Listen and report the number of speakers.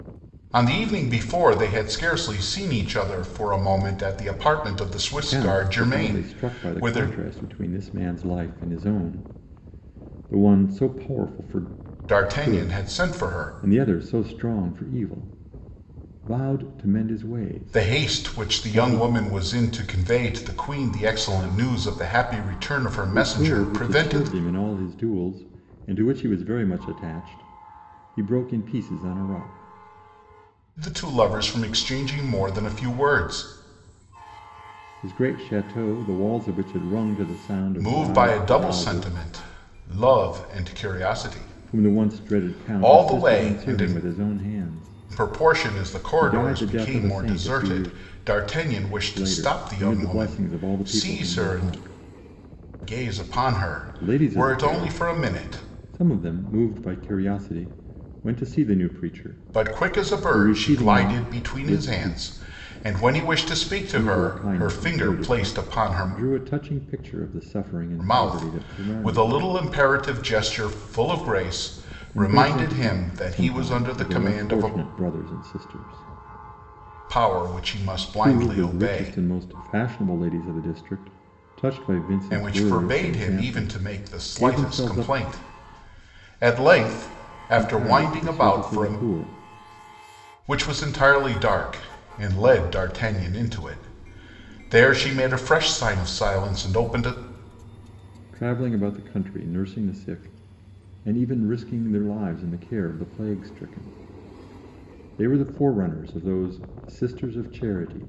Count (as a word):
two